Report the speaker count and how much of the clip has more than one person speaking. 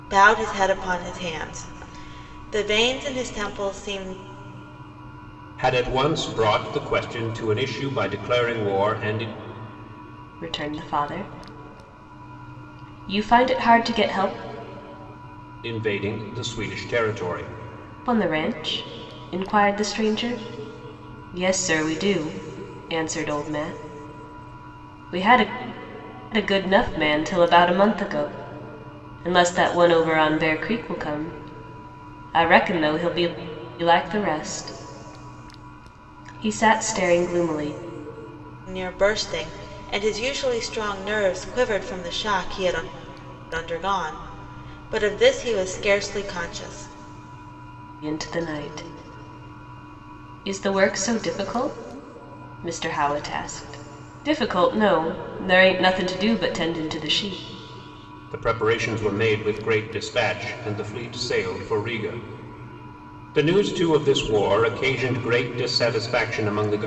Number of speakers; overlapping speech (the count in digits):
3, no overlap